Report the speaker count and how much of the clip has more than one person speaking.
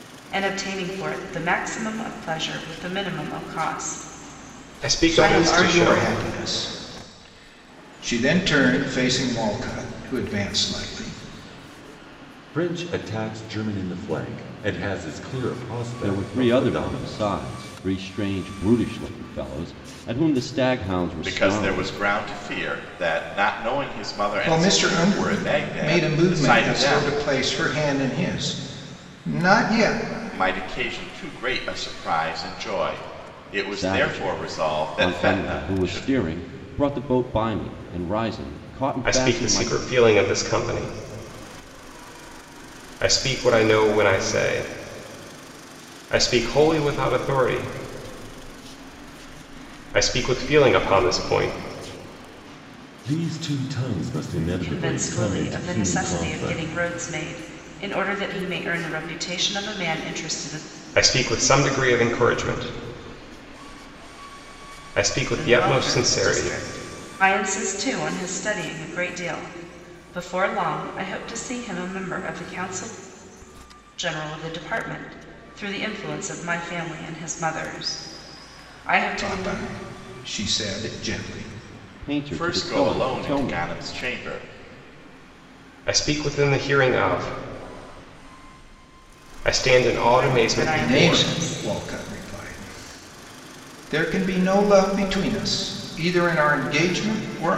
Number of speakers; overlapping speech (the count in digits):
6, about 17%